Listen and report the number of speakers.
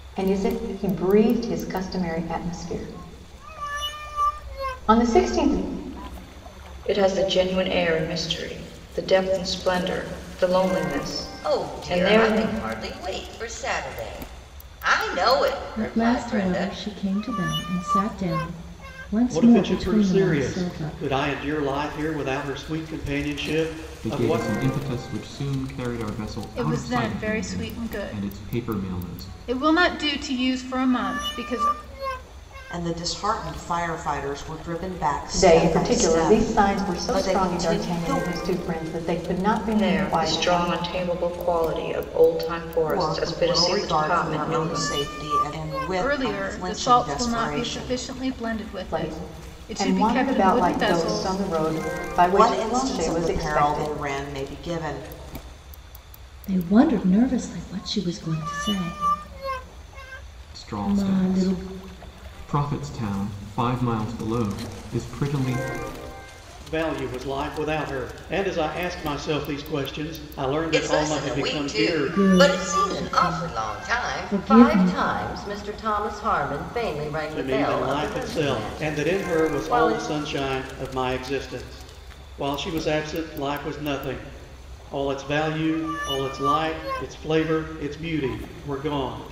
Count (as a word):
eight